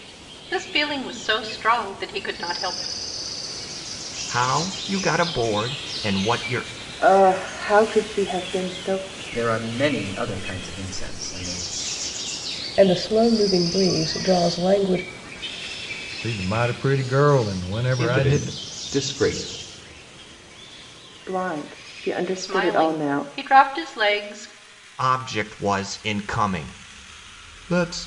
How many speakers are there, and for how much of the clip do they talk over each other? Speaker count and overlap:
7, about 5%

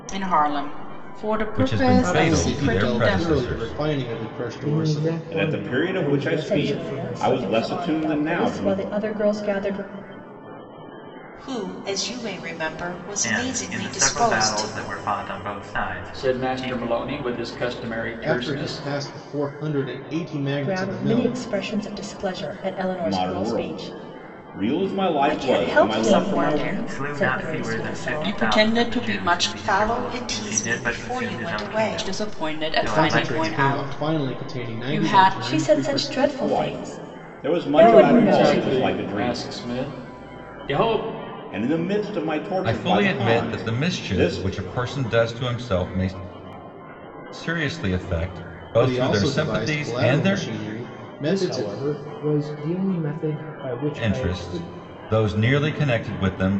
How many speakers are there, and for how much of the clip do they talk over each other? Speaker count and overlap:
9, about 52%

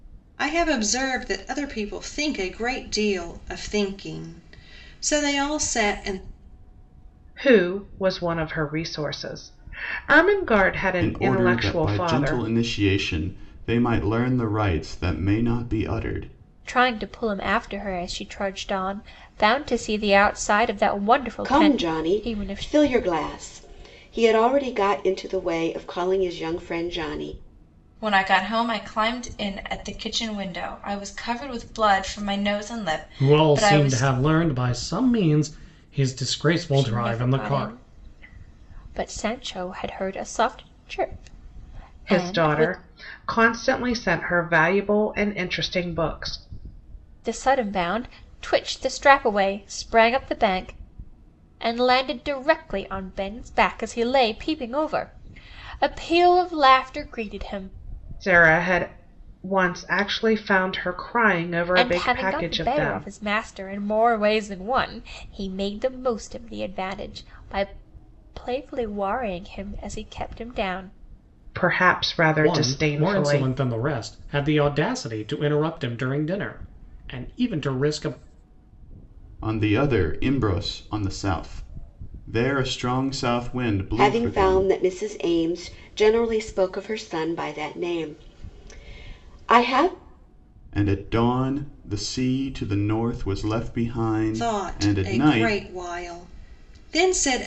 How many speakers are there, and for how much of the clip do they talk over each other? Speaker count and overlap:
7, about 10%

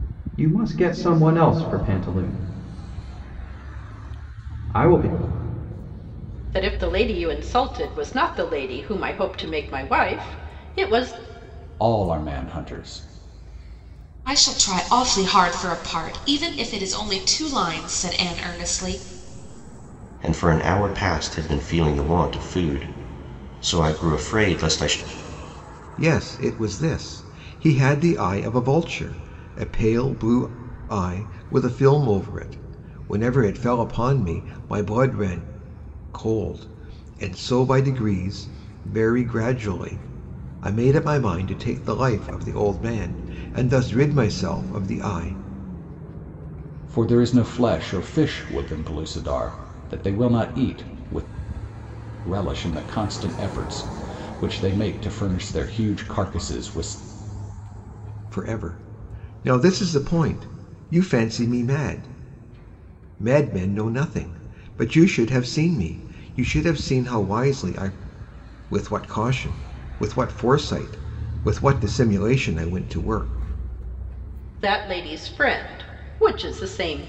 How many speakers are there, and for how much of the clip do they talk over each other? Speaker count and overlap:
6, no overlap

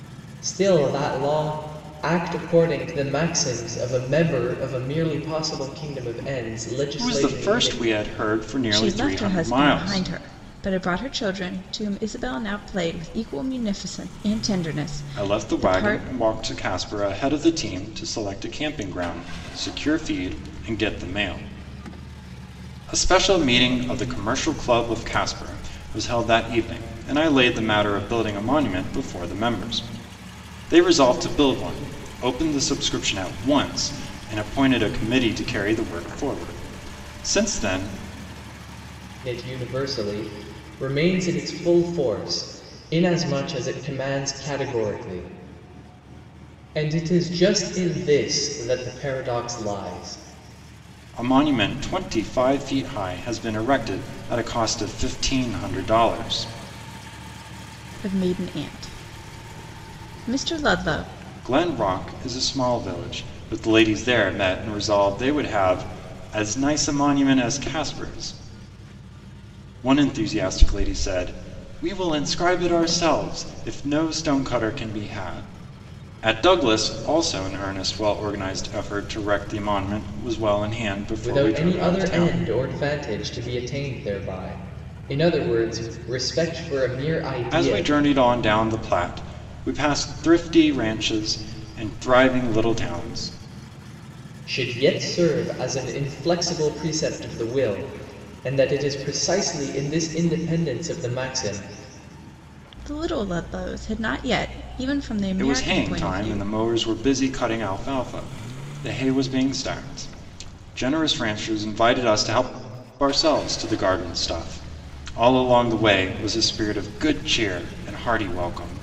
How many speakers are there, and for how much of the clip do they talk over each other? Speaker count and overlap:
3, about 5%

